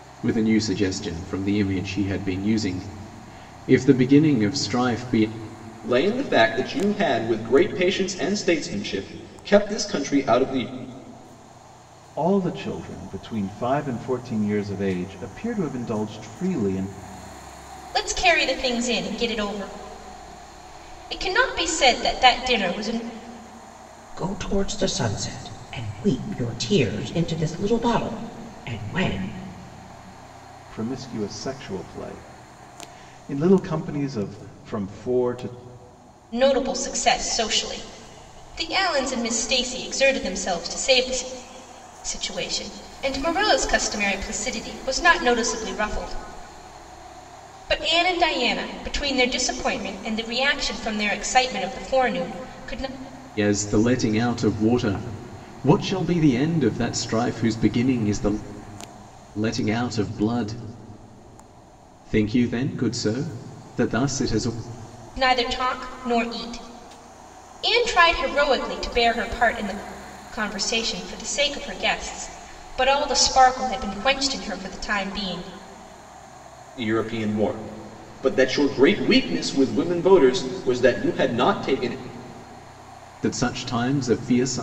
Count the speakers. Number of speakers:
5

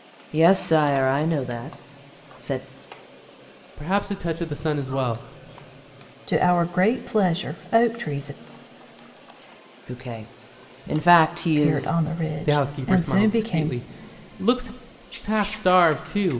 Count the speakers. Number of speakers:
3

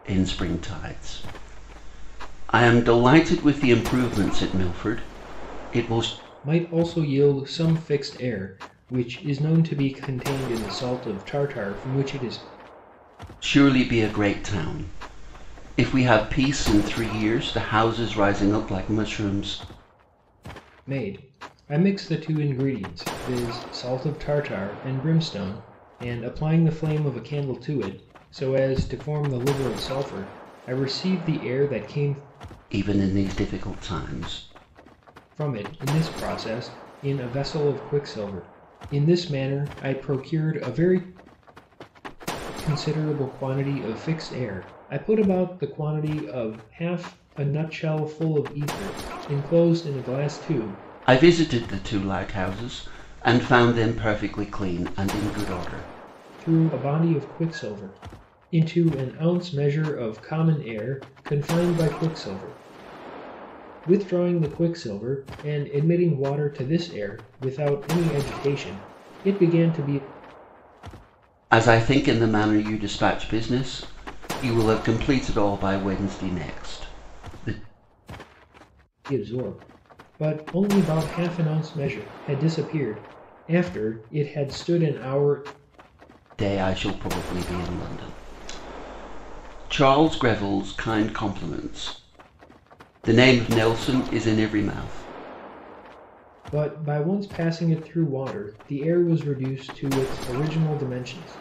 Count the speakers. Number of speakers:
2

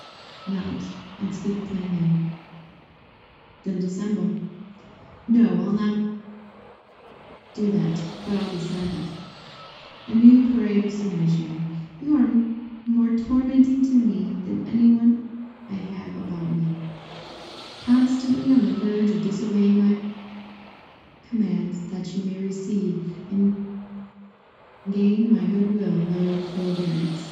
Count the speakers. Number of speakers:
1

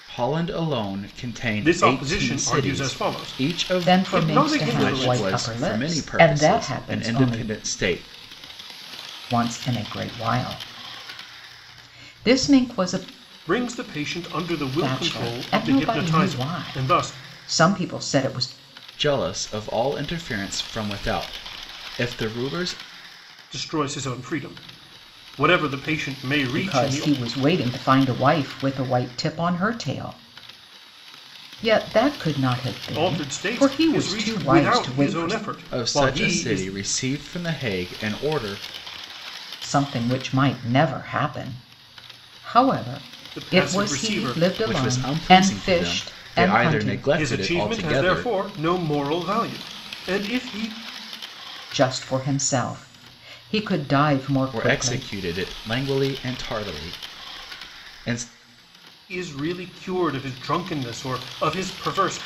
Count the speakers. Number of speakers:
3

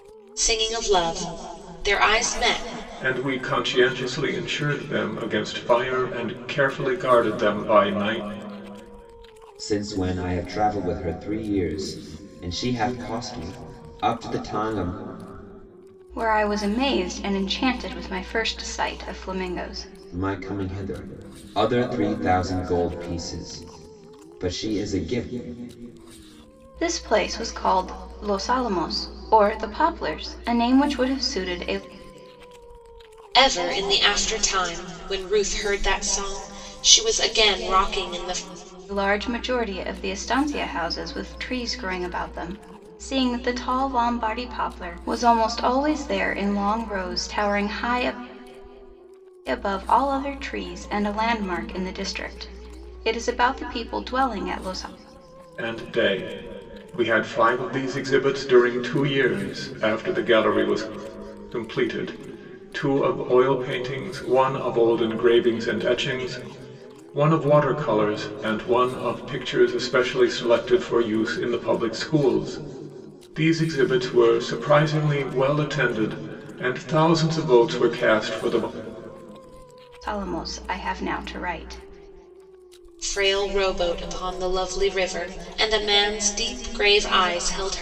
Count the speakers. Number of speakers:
4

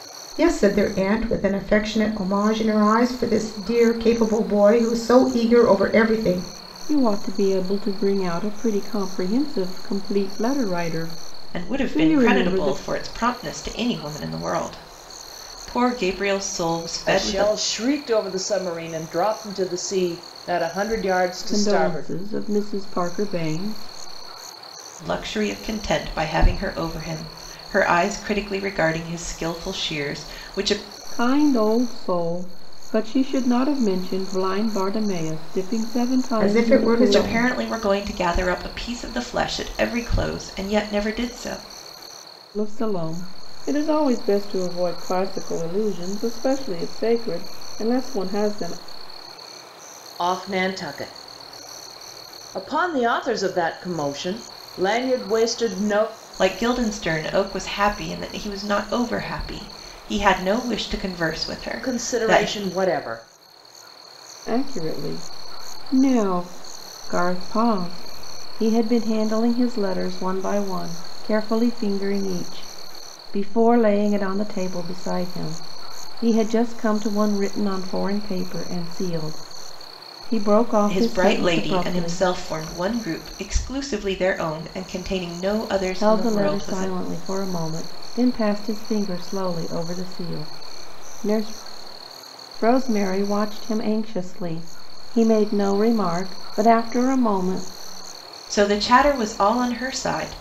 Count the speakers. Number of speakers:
4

